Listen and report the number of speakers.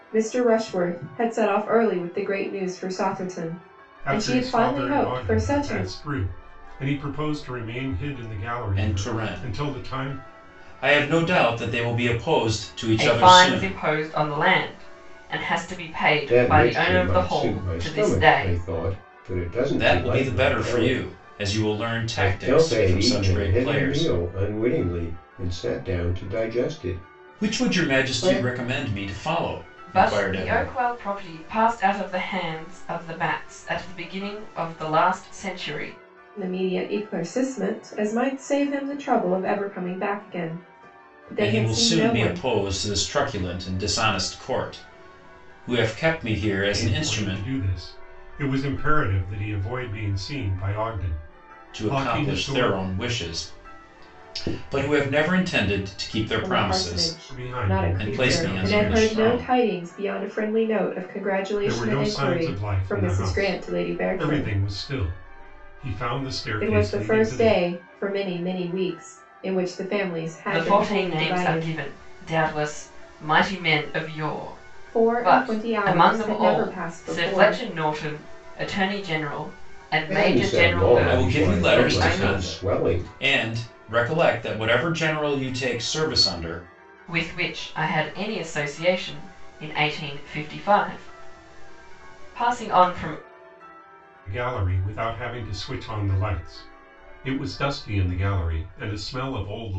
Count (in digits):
5